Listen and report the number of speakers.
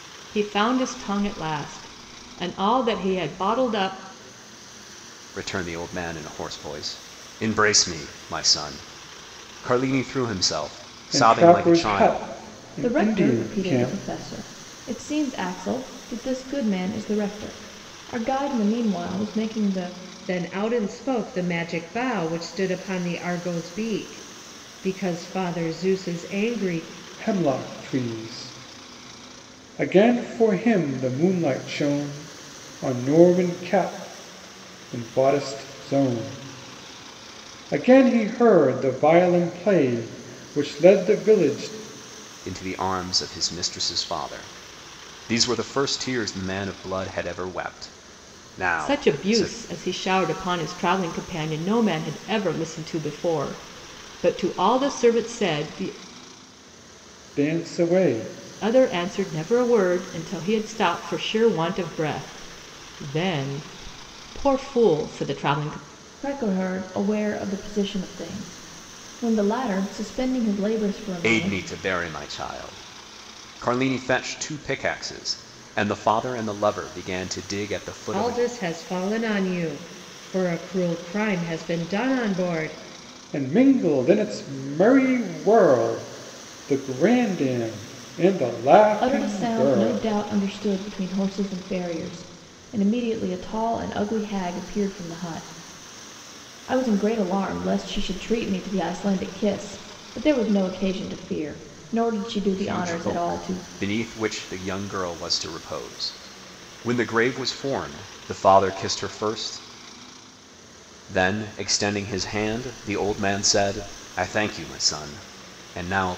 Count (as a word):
five